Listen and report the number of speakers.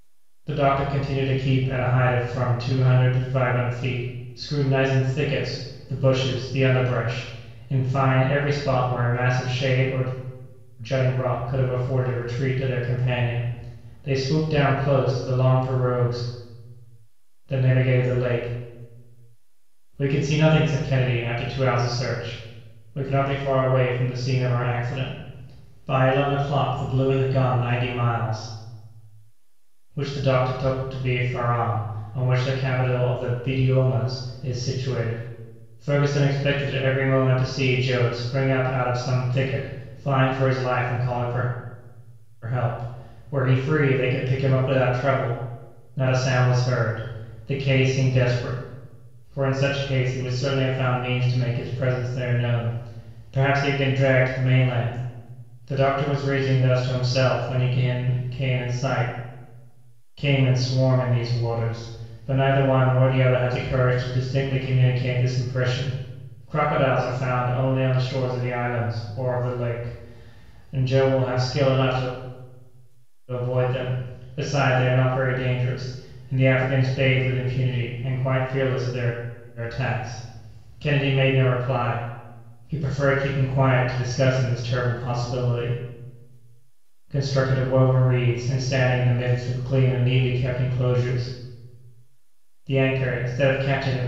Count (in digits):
1